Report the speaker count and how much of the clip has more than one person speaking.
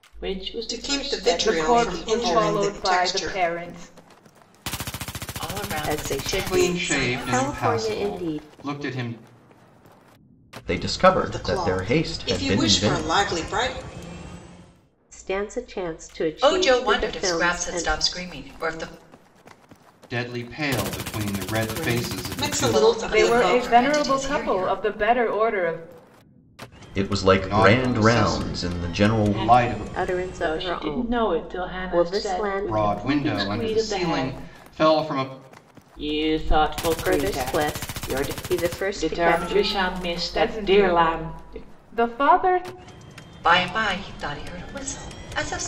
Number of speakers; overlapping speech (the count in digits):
7, about 51%